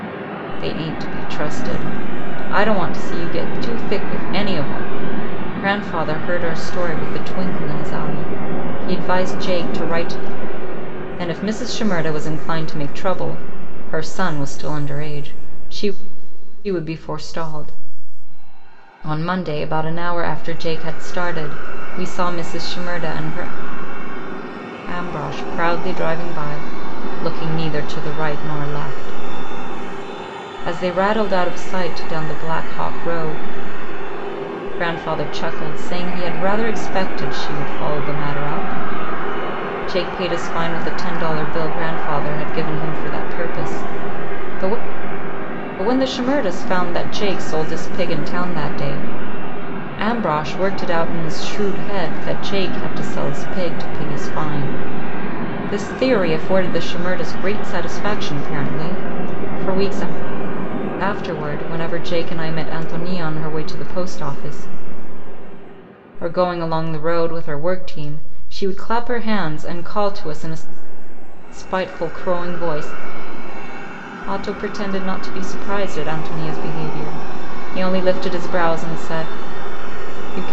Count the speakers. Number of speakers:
one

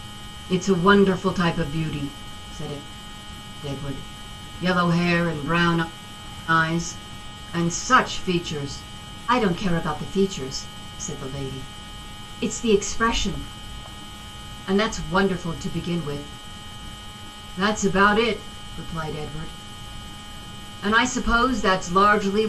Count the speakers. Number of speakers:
one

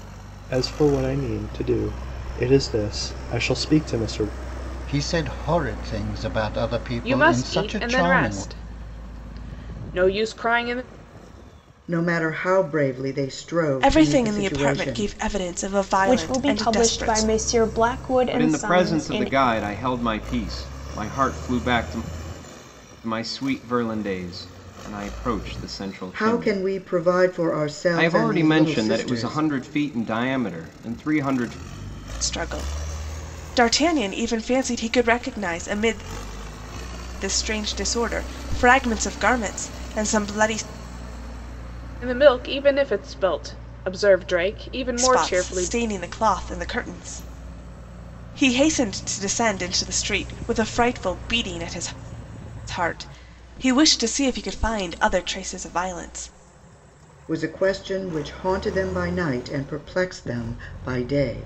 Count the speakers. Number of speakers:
seven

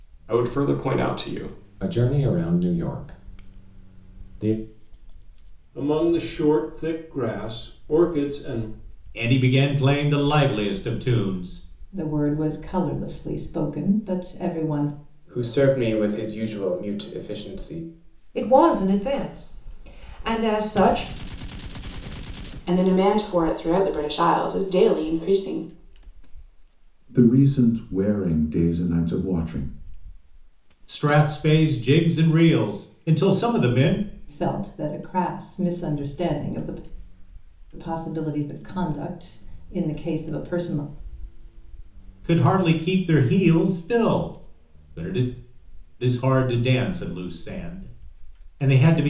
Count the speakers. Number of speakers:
nine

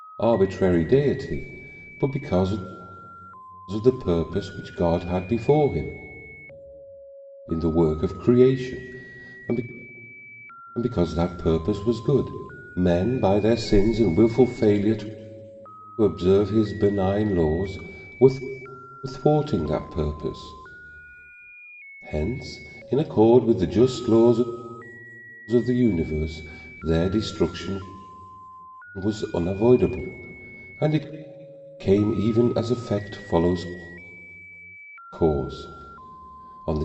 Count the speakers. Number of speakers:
one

